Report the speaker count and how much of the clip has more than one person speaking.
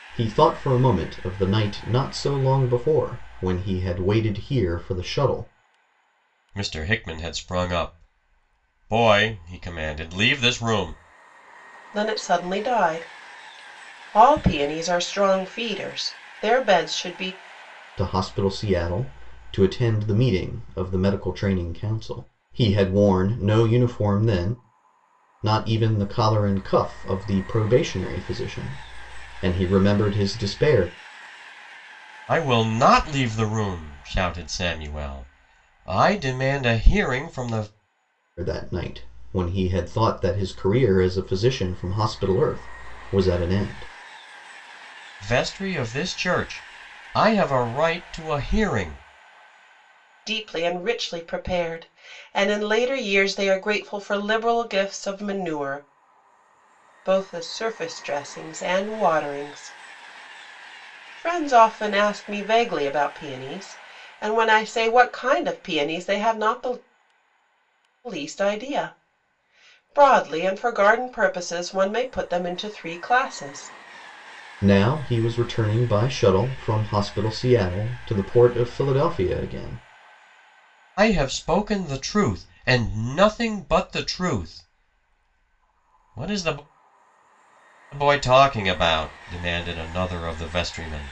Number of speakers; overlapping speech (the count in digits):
3, no overlap